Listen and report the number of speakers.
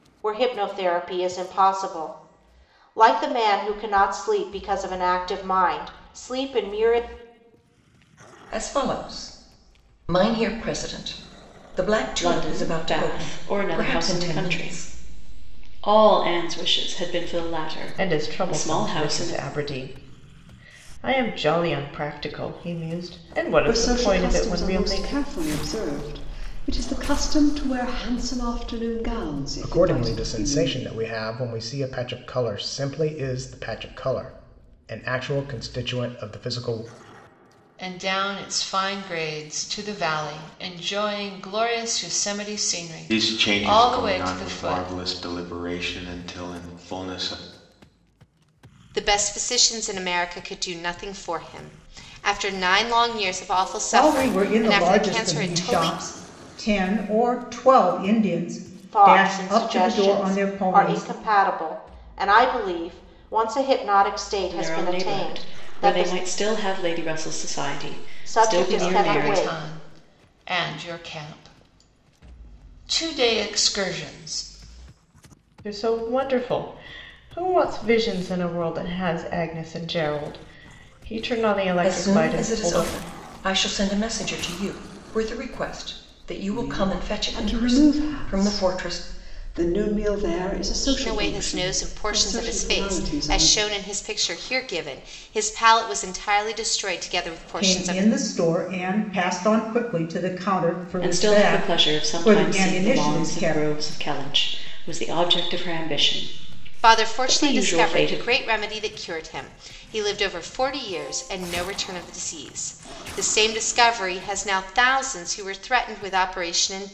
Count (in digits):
10